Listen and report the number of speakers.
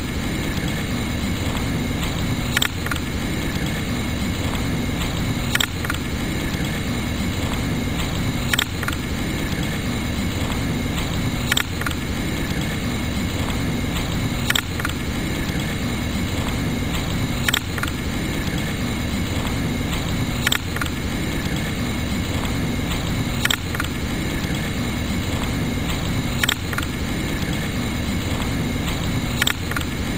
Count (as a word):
zero